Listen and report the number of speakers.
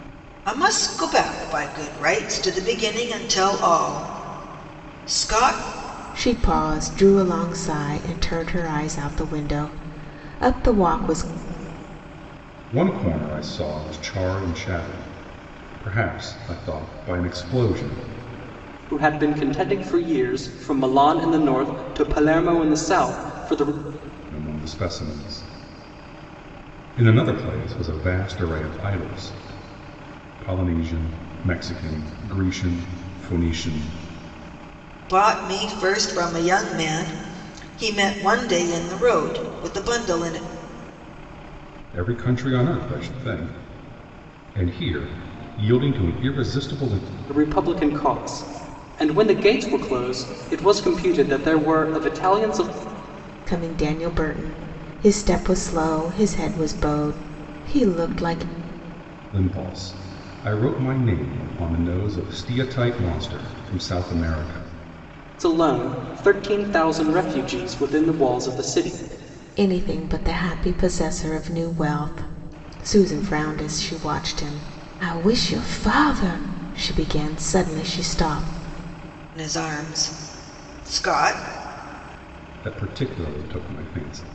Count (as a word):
four